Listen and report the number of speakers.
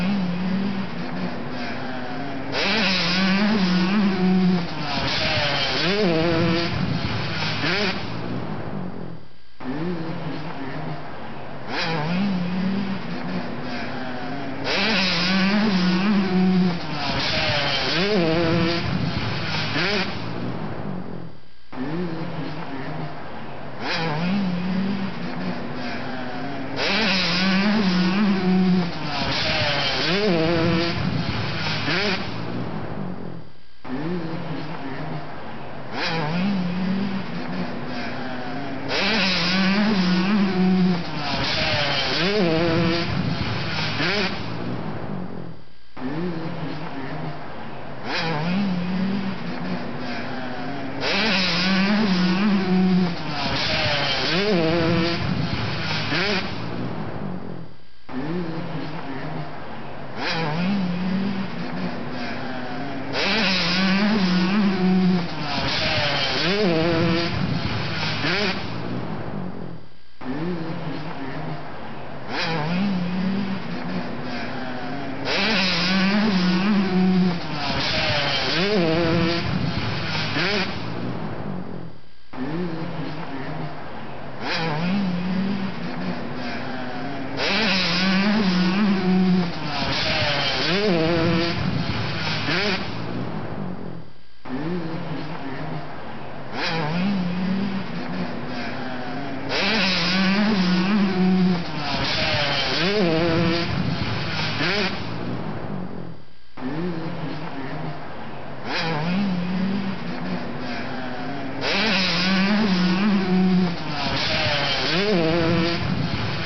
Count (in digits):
0